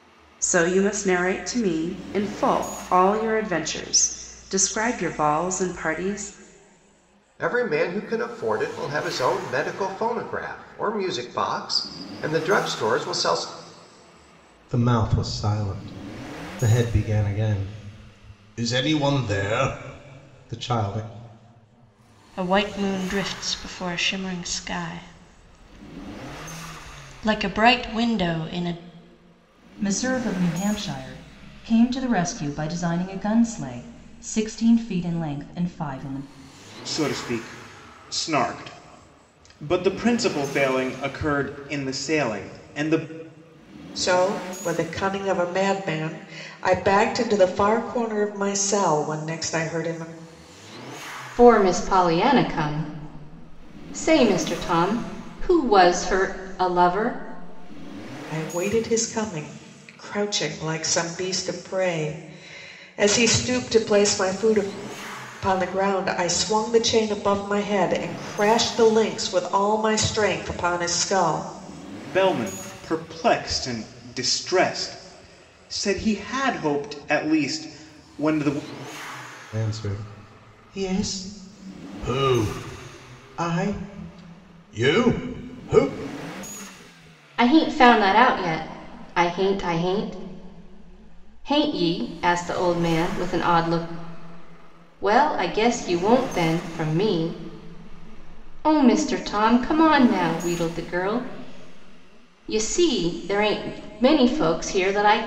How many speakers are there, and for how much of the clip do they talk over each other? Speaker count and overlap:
eight, no overlap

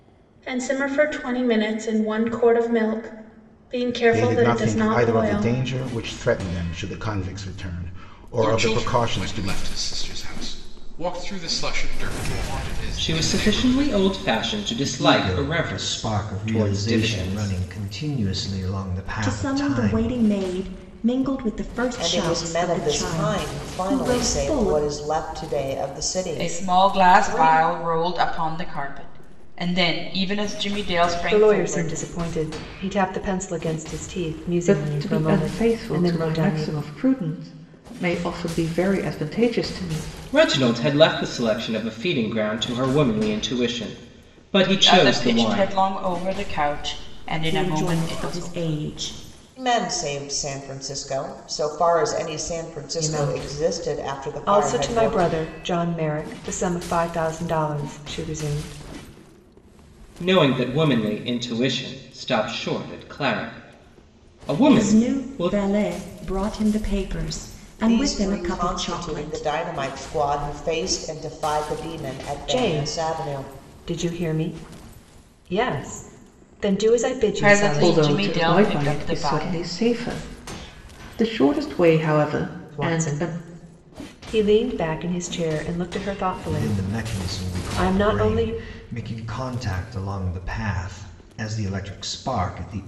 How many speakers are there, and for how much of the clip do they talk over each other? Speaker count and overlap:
ten, about 31%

